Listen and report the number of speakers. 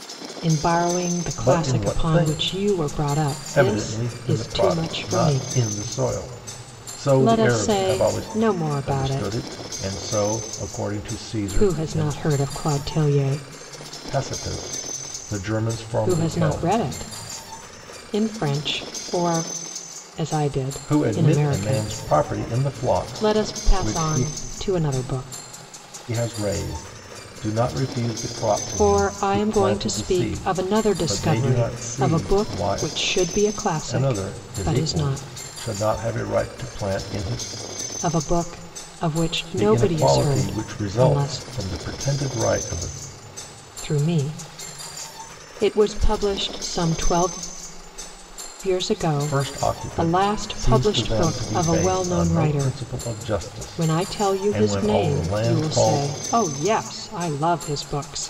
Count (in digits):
2